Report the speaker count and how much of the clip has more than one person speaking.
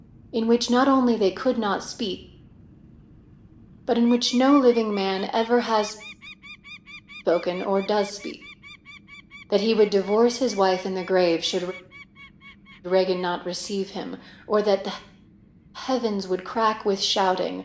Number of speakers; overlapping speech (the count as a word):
one, no overlap